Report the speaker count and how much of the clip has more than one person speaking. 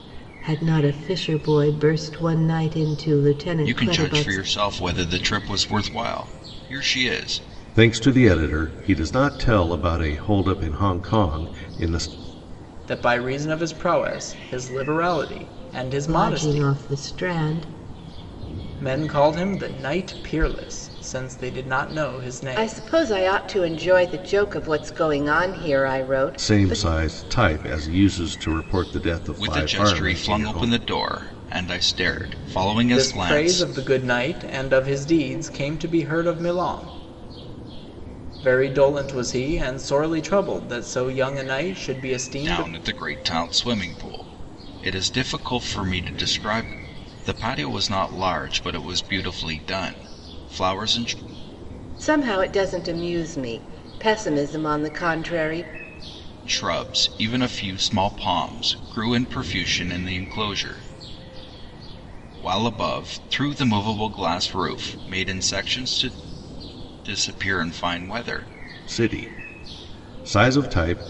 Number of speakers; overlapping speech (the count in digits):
4, about 7%